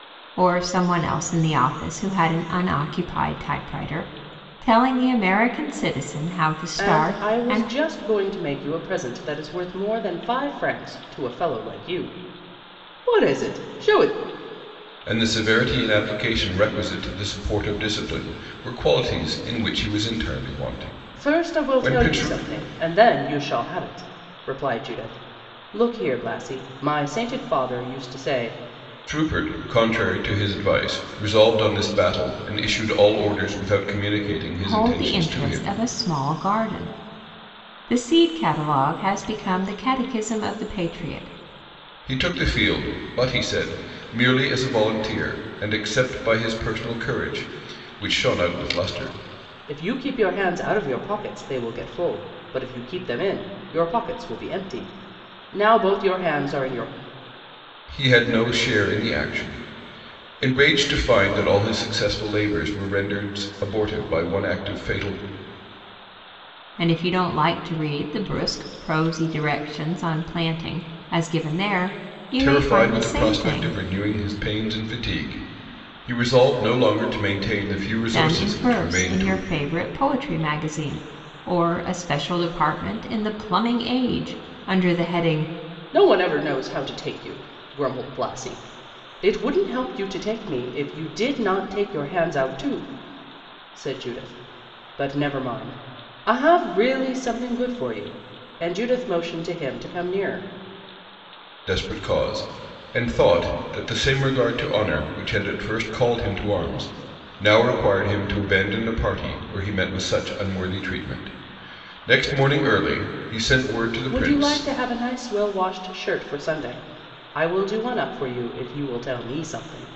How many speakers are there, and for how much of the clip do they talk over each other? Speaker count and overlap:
3, about 6%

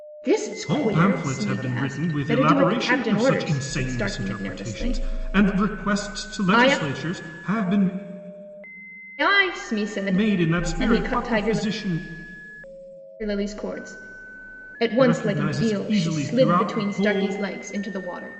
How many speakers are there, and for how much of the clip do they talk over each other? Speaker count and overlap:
2, about 55%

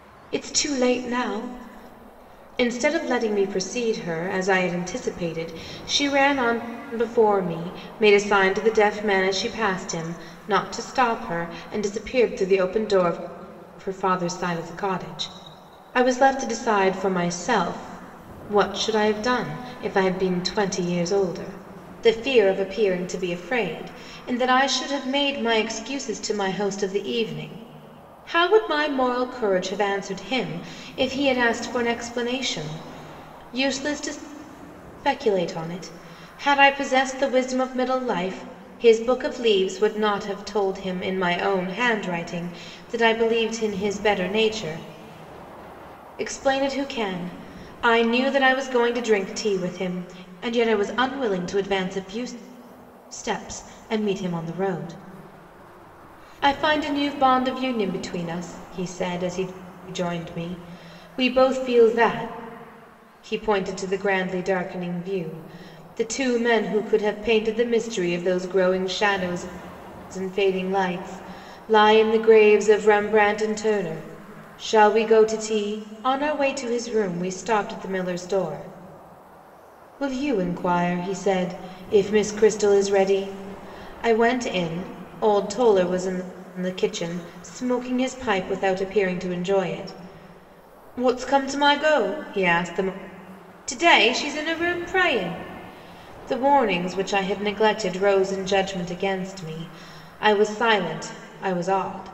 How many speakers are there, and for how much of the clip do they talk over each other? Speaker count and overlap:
1, no overlap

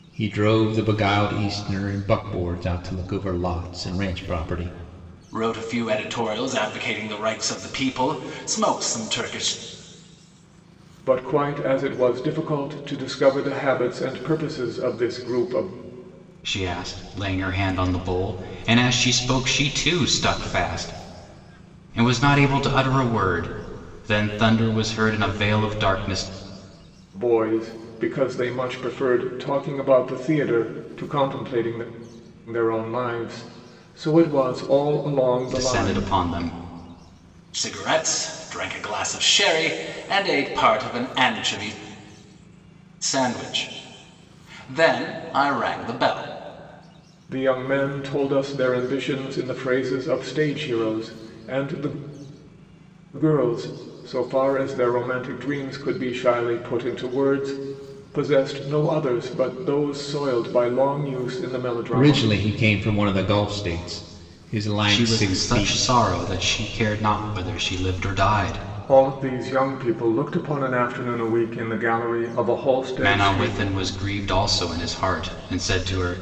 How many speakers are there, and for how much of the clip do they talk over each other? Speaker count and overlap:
4, about 4%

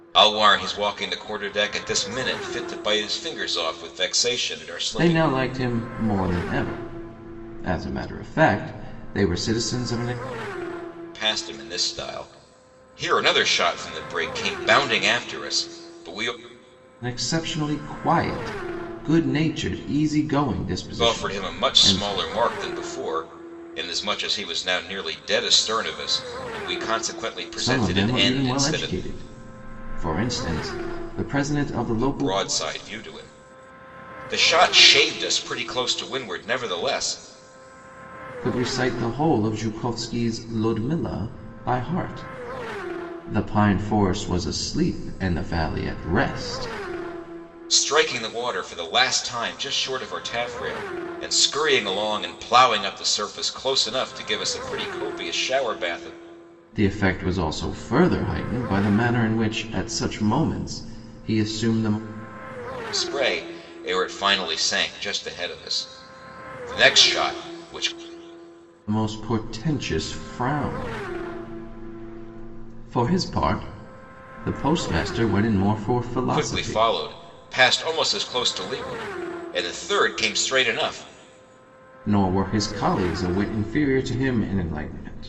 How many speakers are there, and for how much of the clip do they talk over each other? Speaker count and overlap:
2, about 5%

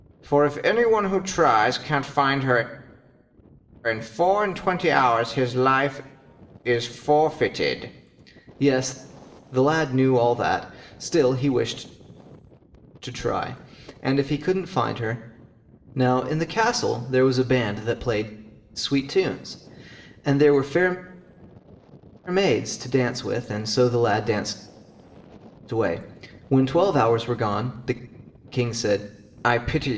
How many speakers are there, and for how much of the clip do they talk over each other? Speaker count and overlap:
1, no overlap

